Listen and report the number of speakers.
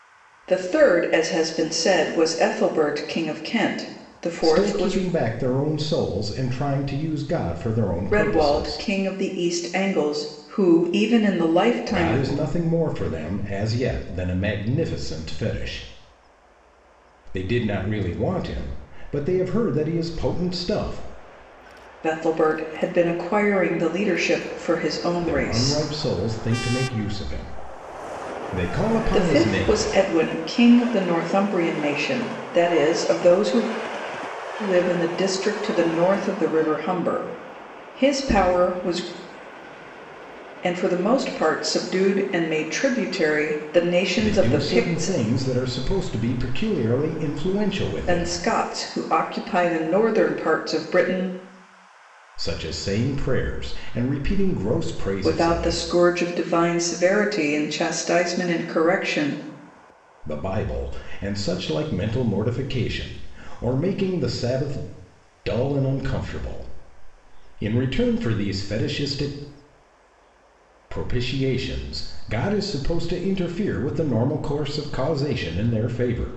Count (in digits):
2